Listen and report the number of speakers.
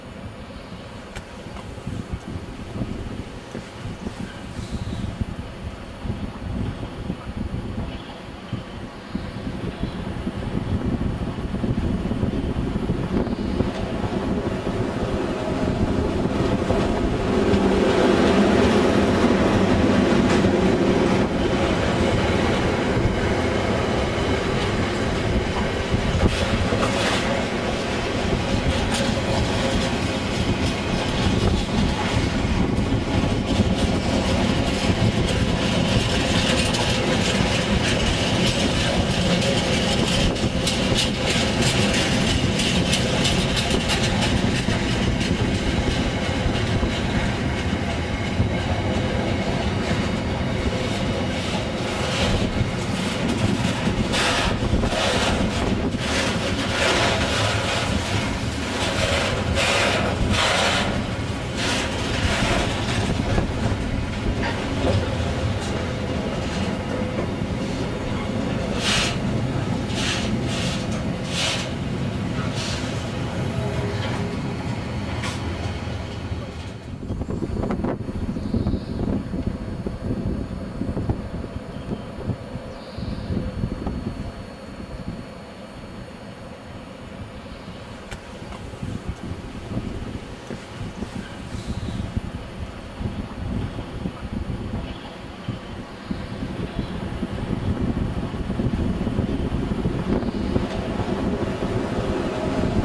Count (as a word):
zero